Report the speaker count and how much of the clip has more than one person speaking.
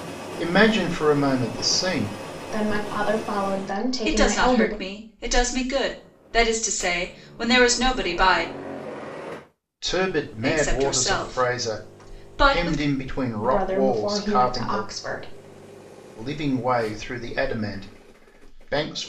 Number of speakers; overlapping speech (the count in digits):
3, about 23%